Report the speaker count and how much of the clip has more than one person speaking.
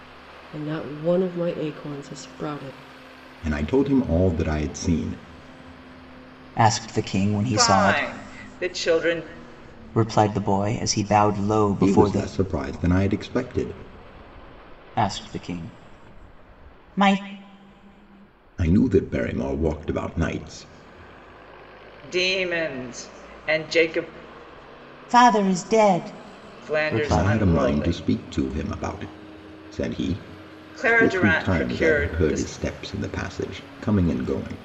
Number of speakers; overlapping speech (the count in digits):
4, about 13%